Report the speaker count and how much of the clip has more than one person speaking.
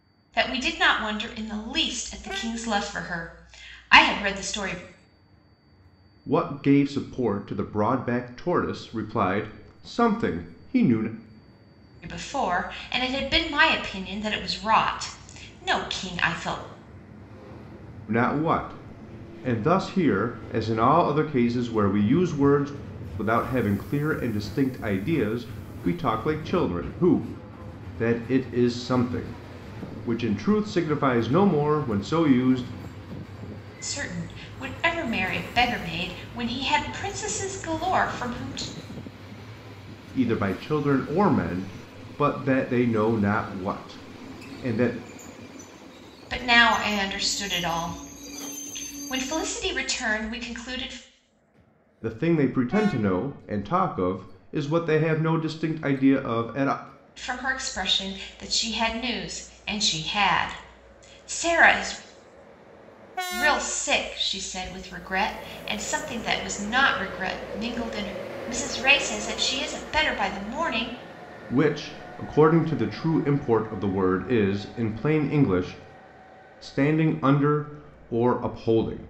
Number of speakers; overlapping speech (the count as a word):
two, no overlap